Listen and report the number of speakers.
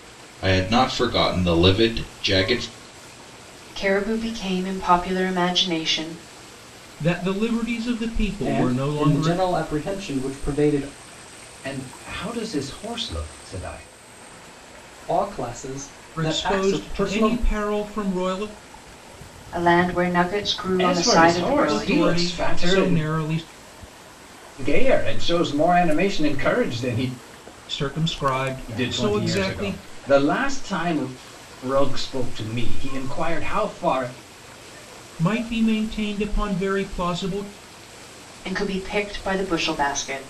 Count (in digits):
5